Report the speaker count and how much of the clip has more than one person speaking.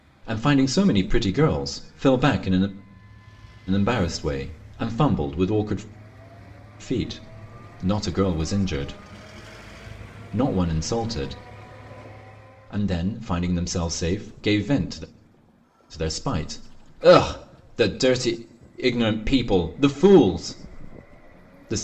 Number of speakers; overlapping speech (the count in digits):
1, no overlap